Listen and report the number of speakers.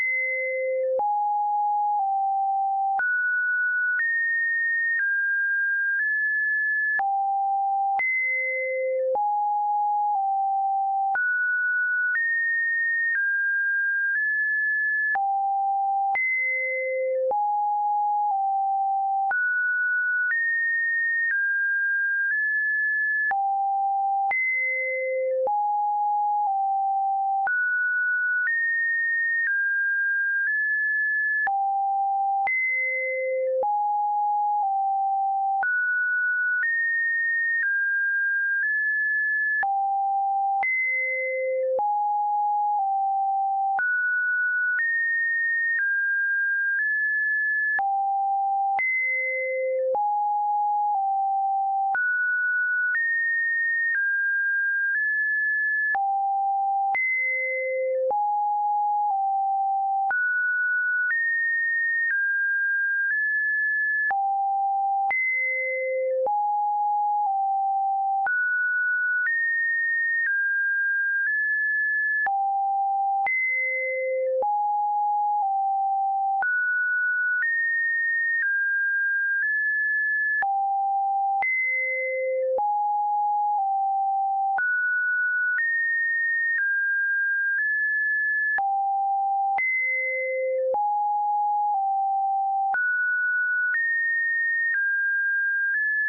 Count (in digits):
0